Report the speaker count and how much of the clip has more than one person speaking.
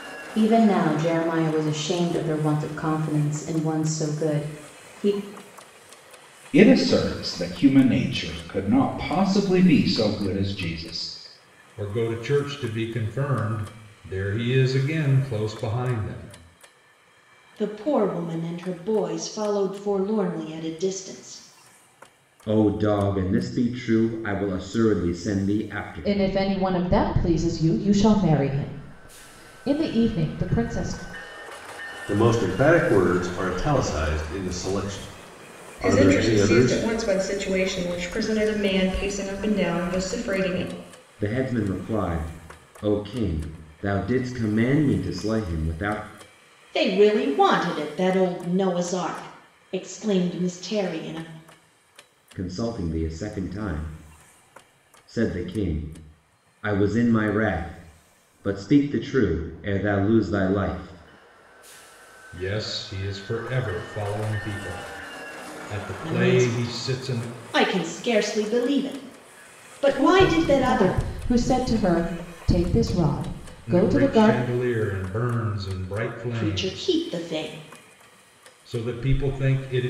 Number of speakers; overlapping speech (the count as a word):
eight, about 7%